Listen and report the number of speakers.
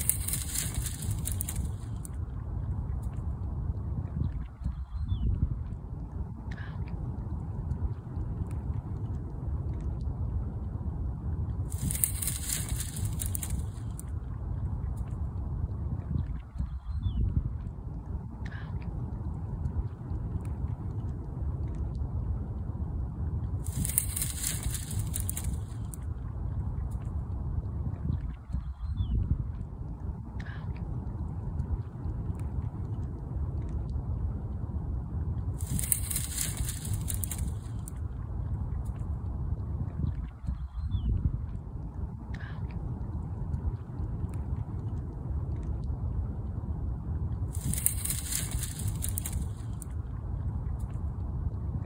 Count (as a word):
zero